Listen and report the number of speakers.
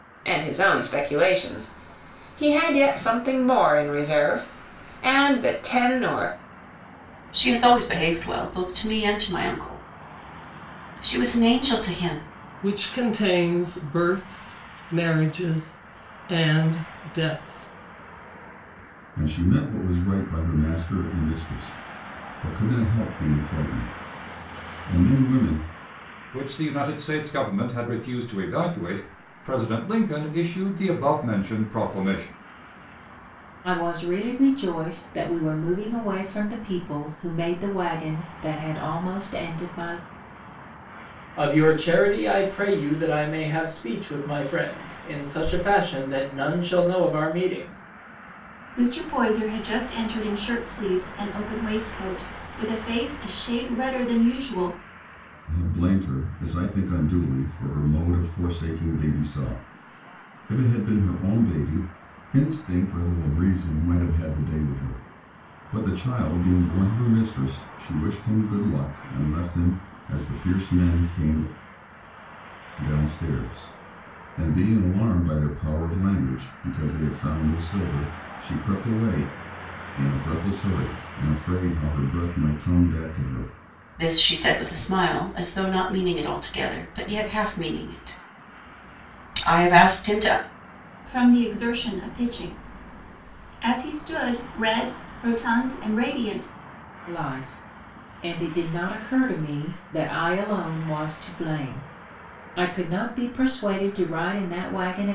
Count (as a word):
eight